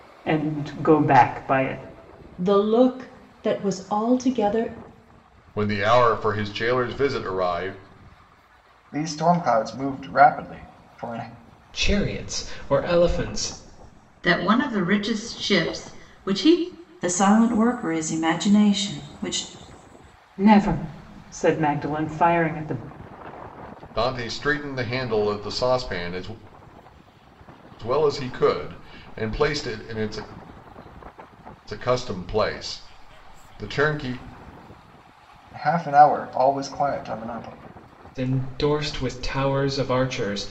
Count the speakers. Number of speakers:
7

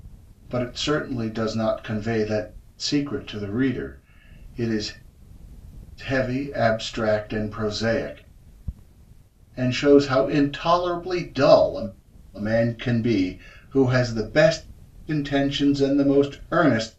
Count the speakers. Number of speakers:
1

